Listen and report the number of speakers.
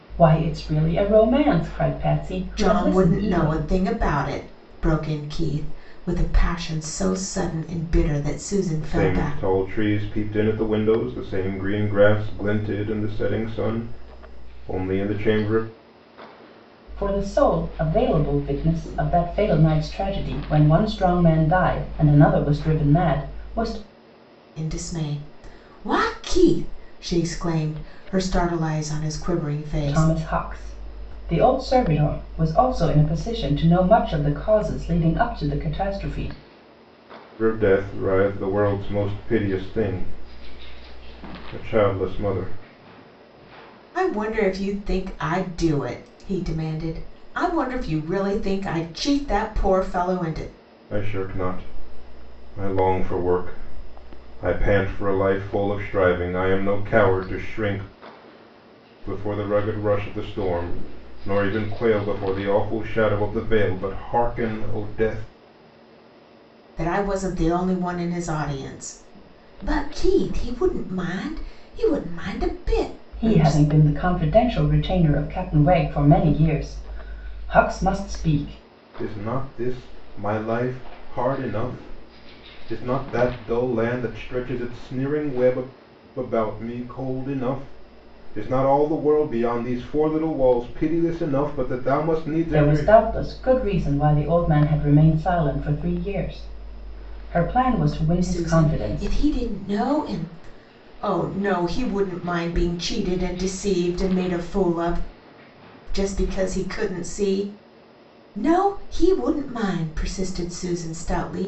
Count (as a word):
three